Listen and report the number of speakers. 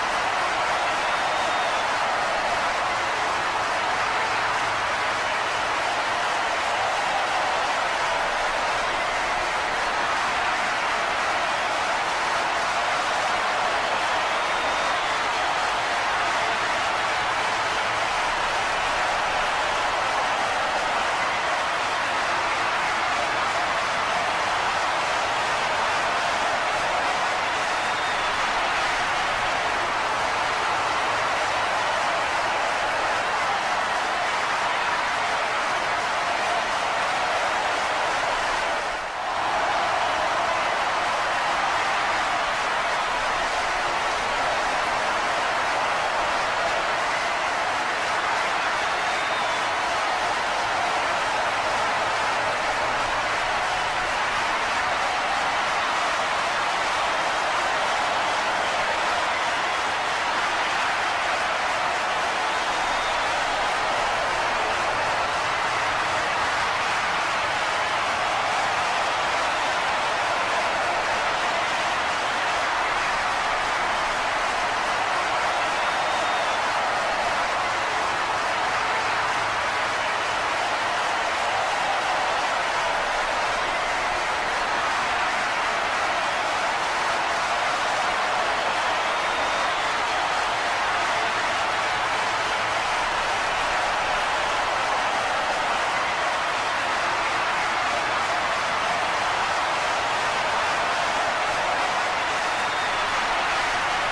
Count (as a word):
zero